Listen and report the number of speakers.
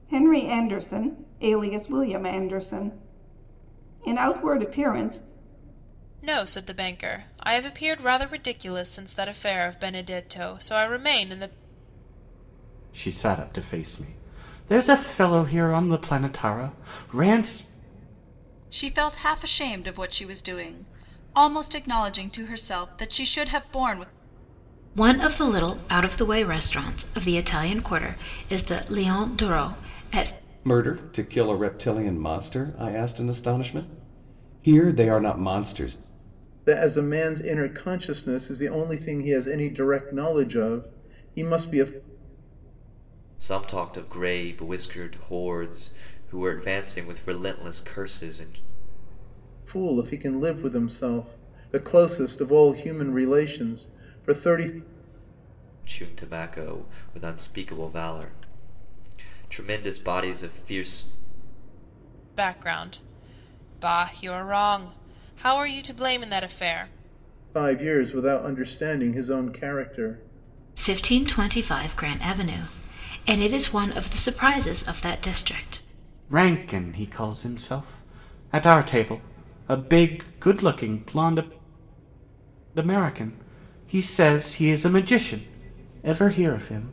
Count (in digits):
8